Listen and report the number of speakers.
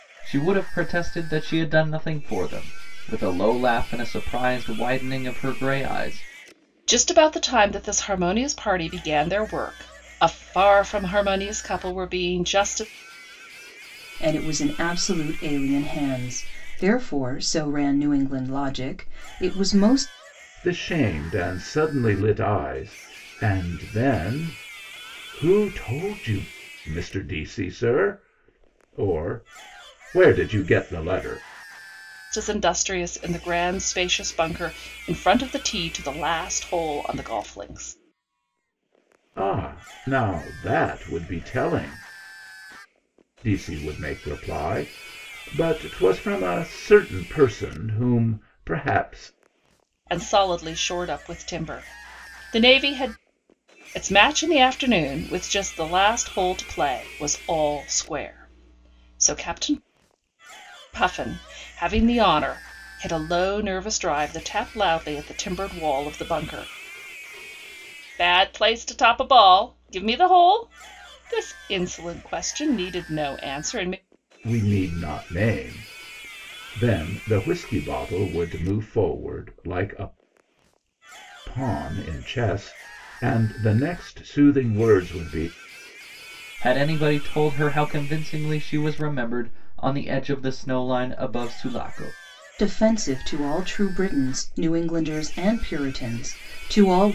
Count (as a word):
four